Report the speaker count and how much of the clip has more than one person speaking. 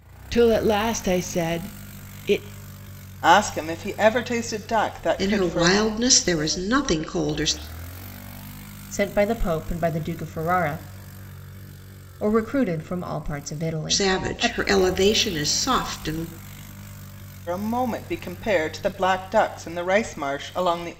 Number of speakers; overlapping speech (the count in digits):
4, about 6%